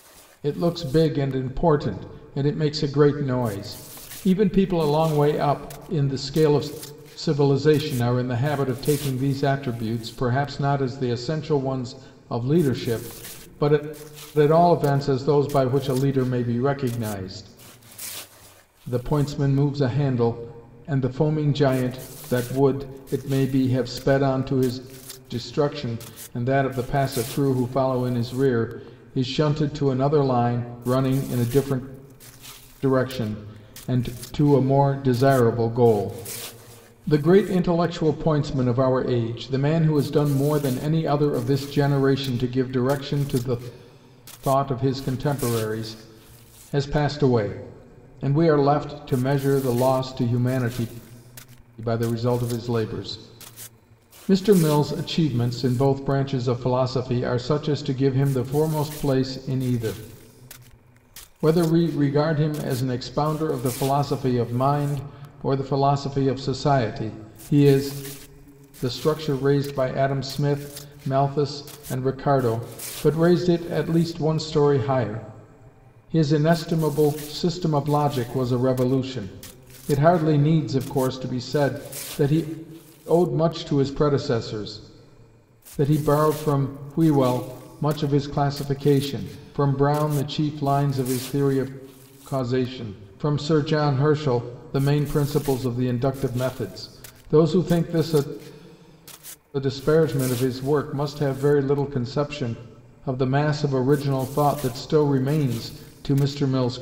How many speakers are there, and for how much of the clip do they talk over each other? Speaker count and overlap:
one, no overlap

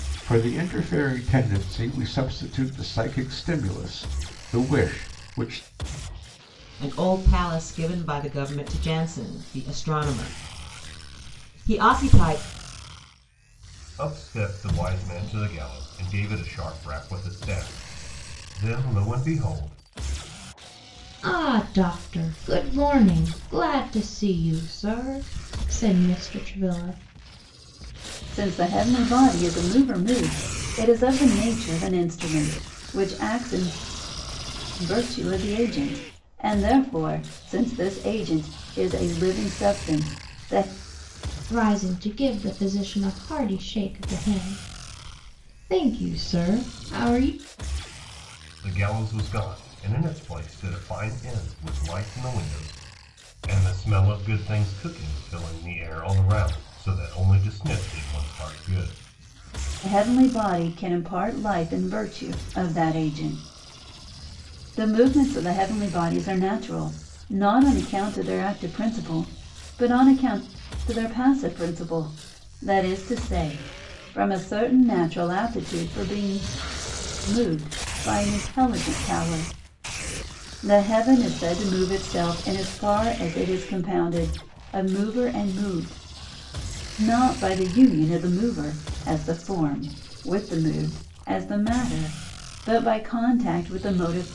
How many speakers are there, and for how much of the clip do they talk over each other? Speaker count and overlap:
five, no overlap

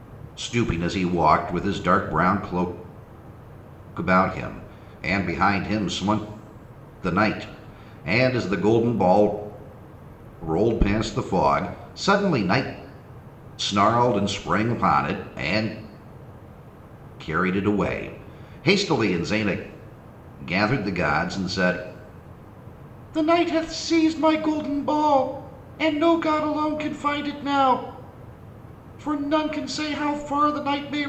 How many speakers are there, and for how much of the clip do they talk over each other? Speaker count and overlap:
one, no overlap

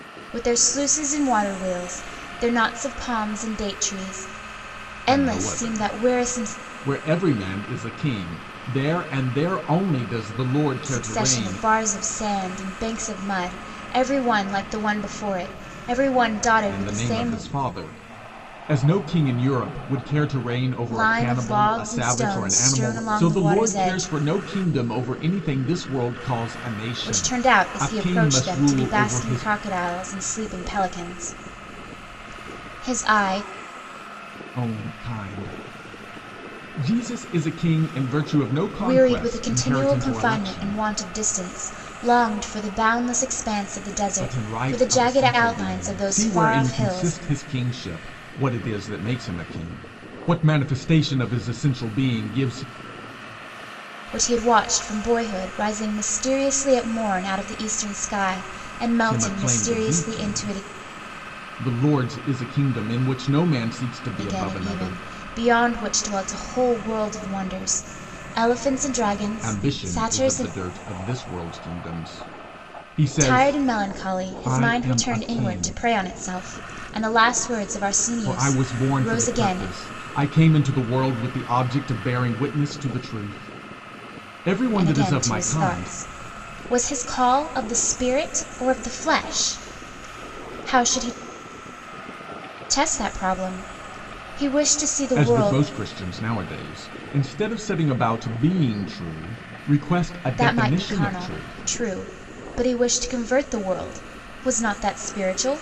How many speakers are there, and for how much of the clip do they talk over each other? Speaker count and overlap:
two, about 23%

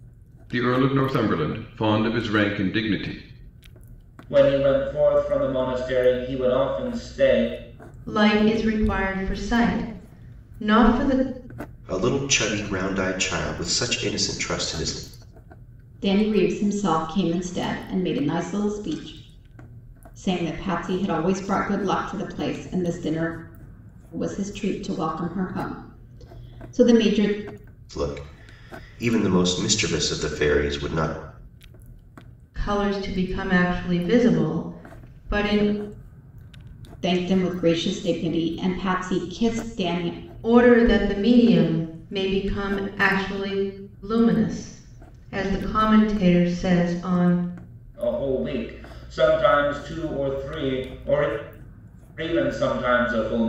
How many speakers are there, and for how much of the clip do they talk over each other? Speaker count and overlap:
five, no overlap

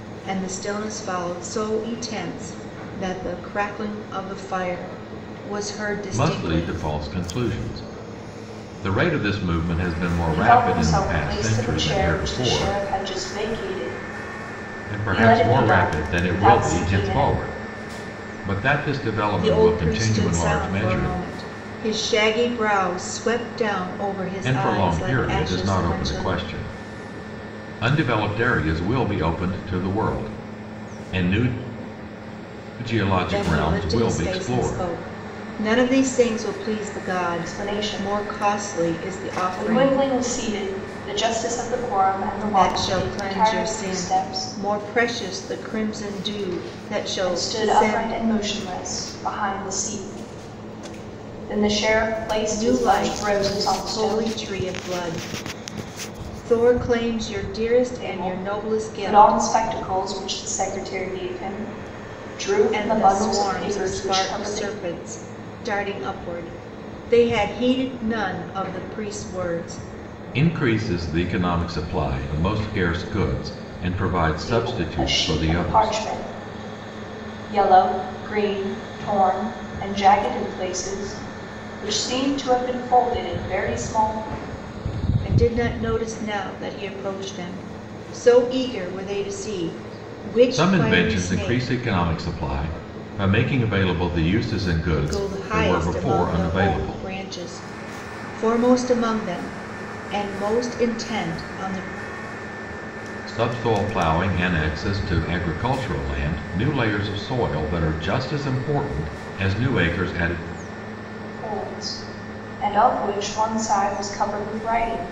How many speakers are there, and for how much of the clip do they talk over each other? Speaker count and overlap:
three, about 24%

